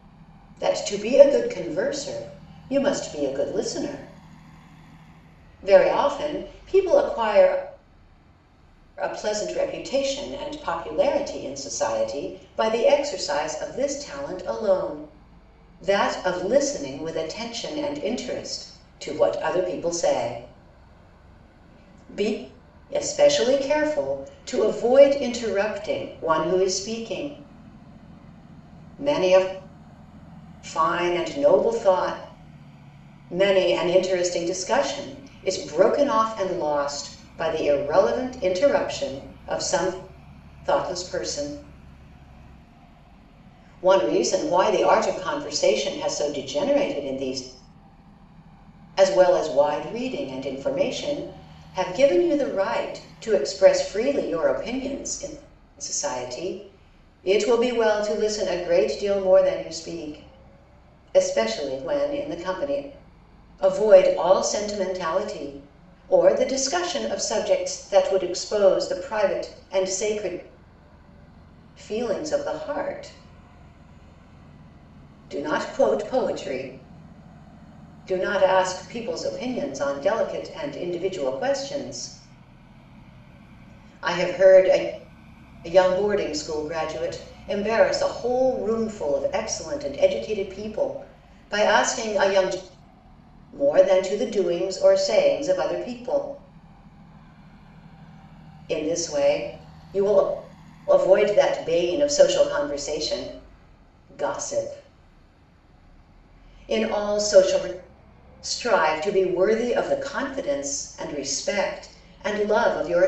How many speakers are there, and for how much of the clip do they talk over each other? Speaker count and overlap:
1, no overlap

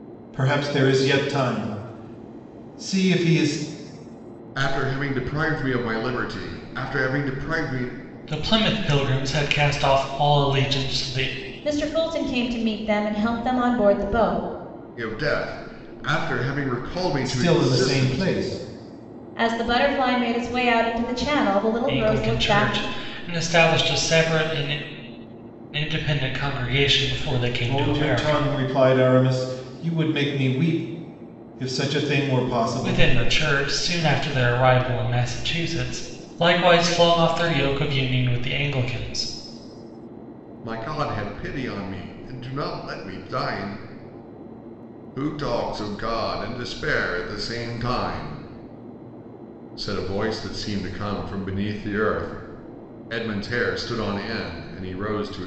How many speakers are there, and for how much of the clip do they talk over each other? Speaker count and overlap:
4, about 6%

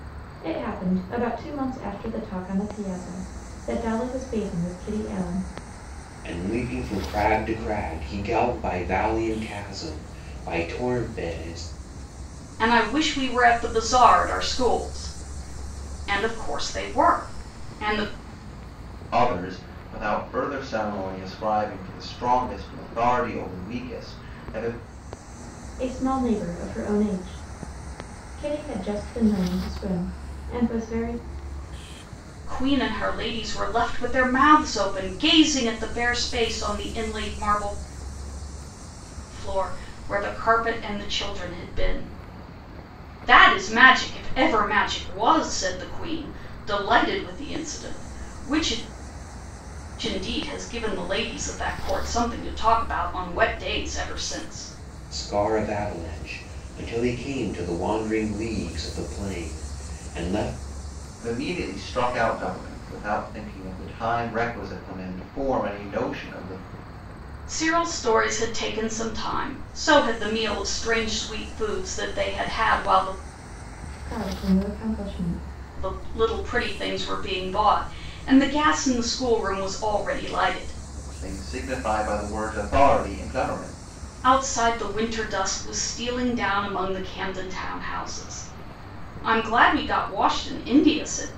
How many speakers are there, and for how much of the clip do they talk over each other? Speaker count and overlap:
4, no overlap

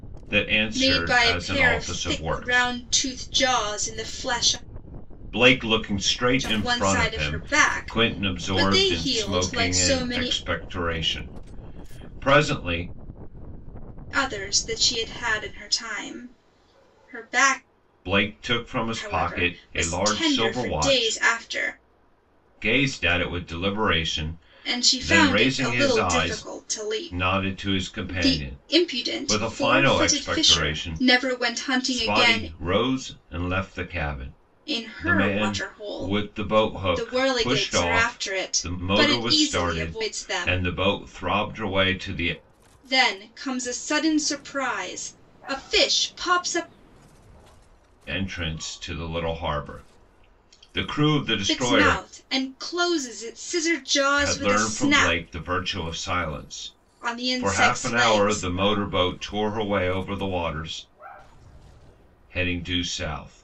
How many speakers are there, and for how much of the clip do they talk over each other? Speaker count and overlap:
2, about 35%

